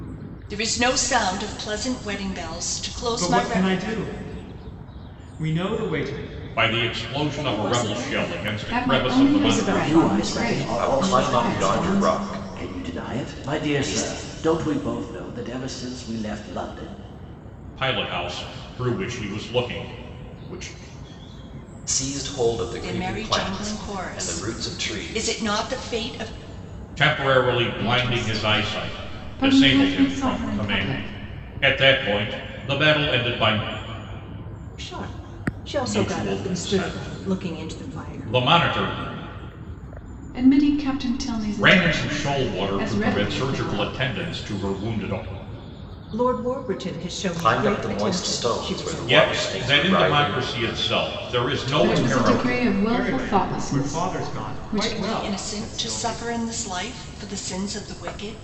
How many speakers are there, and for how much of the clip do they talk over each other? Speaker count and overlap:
7, about 46%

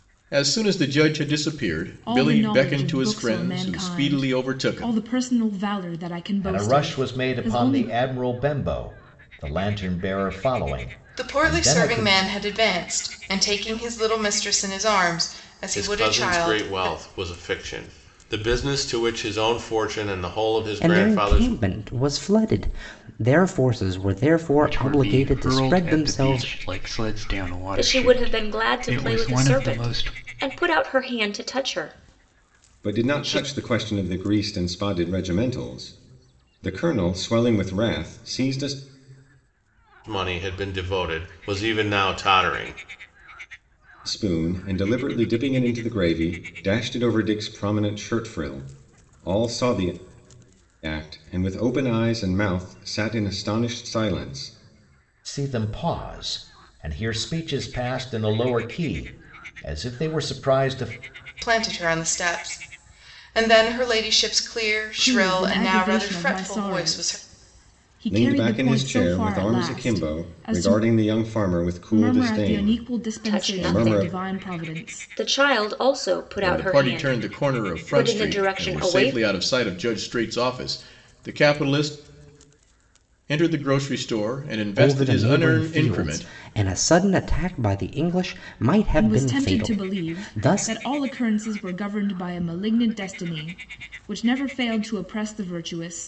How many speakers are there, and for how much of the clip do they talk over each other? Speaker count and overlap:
9, about 28%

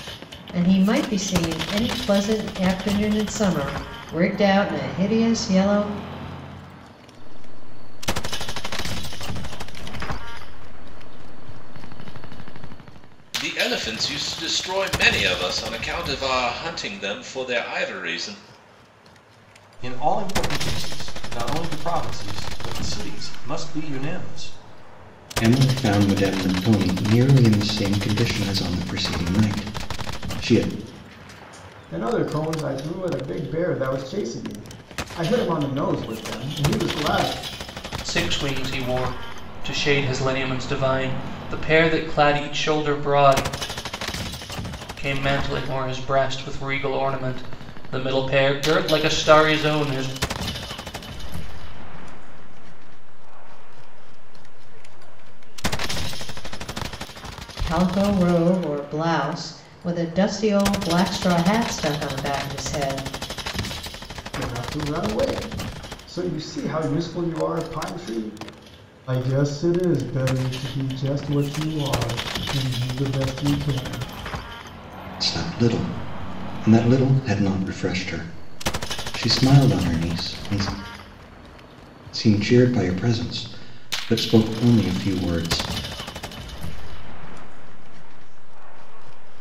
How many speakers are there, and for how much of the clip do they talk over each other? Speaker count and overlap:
7, no overlap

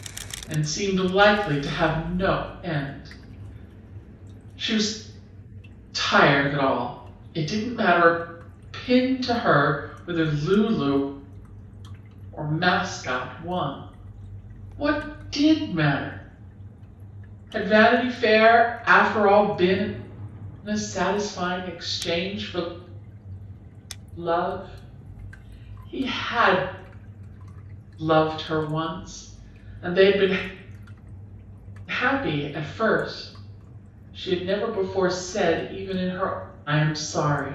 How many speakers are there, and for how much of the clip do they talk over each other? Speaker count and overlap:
1, no overlap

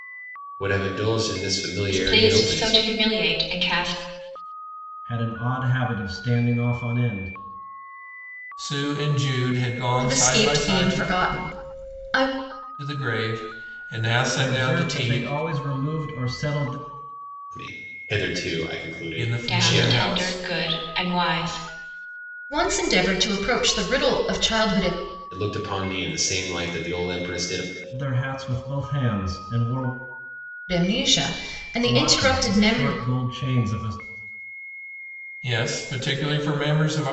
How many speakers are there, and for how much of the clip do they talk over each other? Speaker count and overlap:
5, about 15%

